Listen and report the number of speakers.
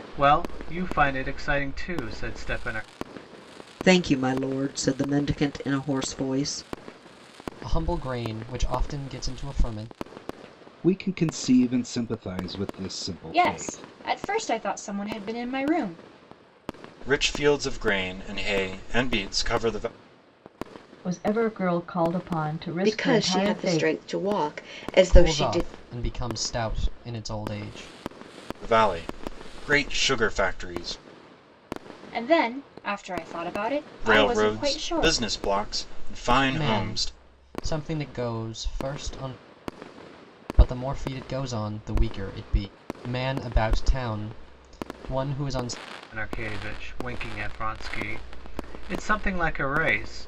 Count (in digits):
8